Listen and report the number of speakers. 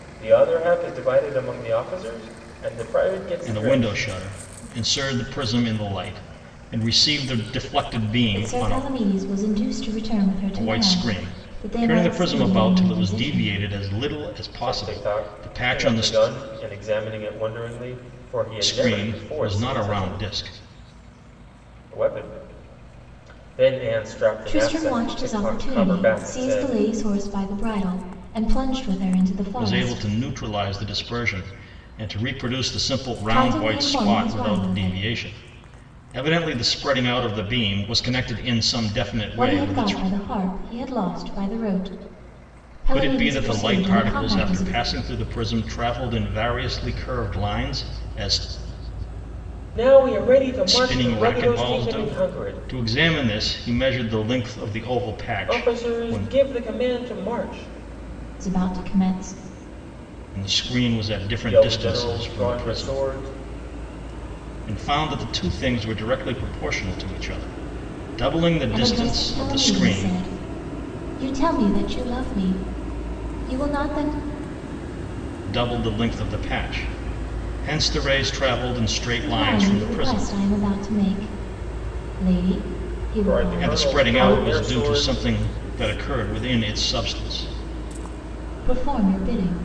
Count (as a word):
three